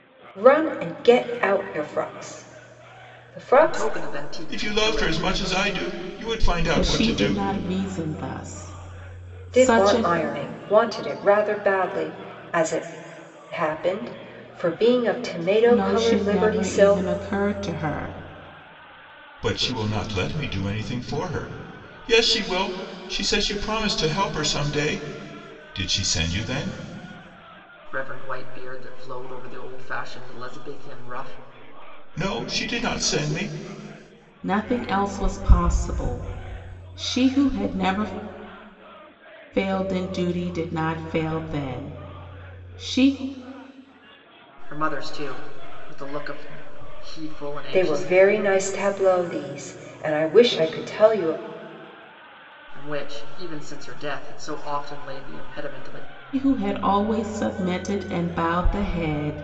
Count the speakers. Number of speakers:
4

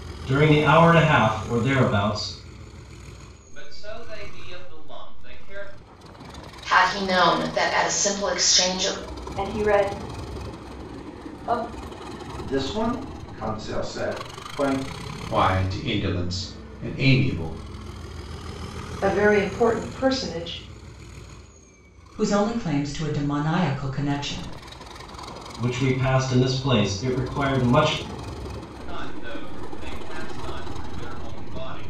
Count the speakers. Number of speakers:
8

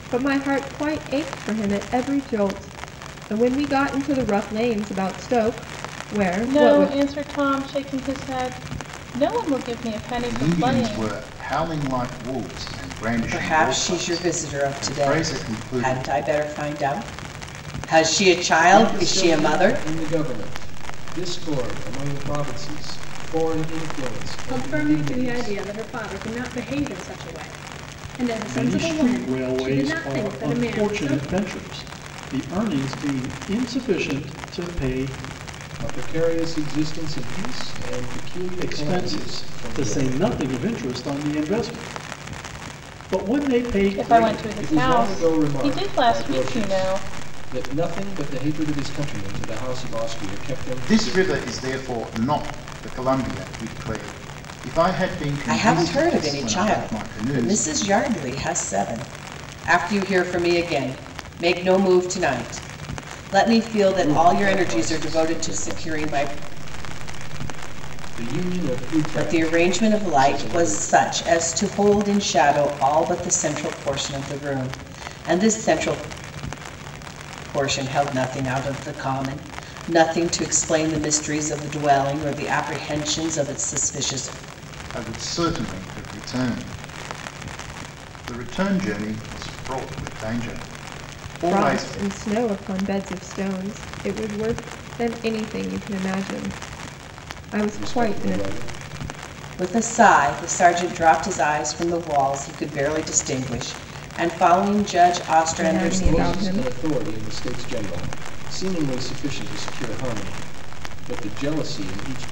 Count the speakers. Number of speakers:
7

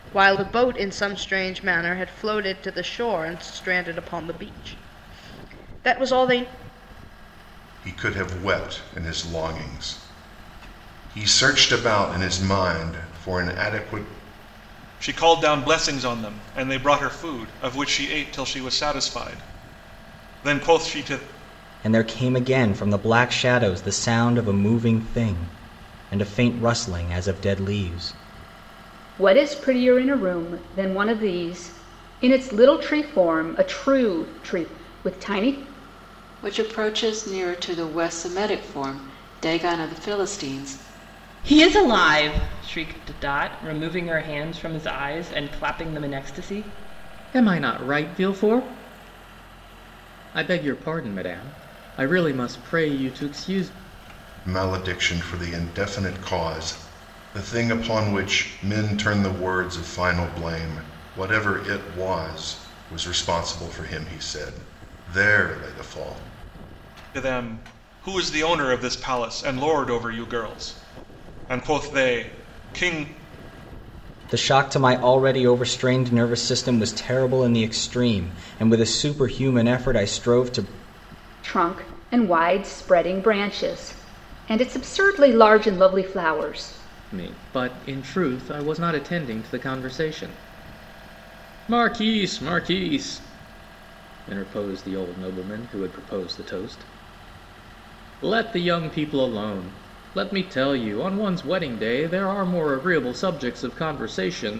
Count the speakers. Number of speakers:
8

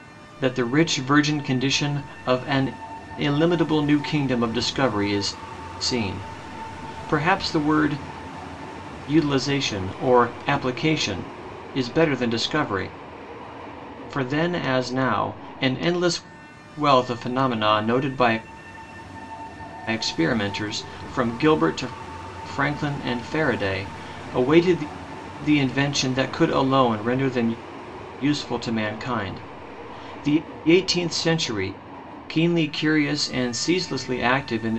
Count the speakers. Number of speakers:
1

